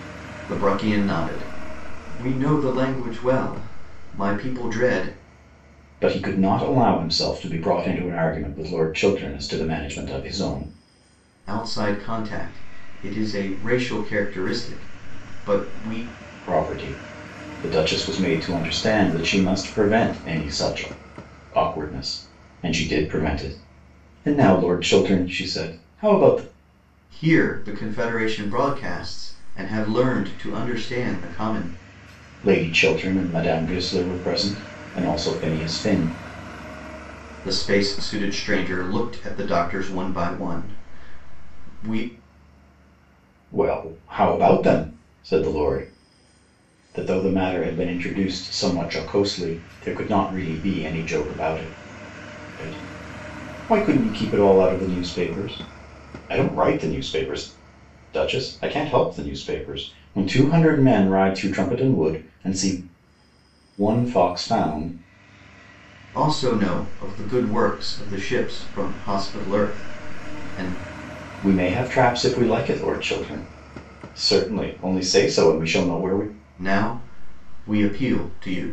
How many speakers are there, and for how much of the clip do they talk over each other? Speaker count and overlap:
2, no overlap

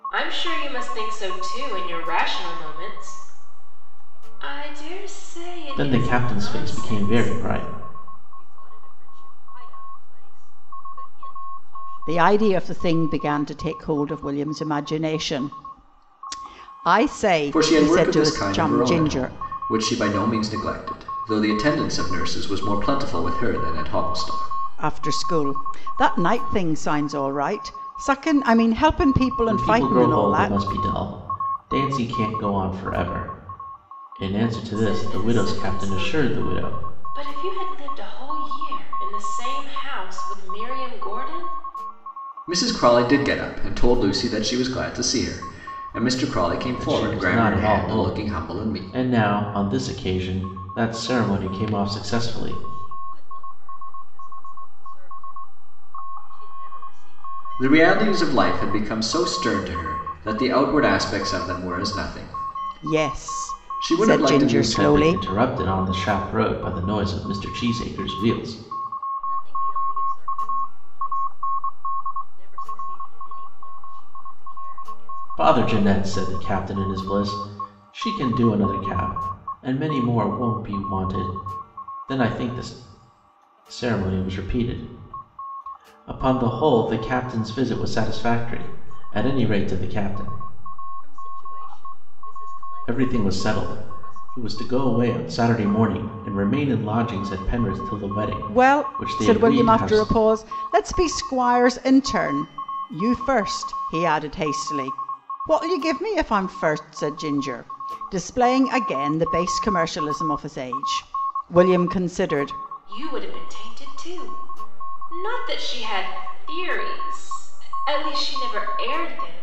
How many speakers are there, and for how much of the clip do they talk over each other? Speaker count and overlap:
5, about 23%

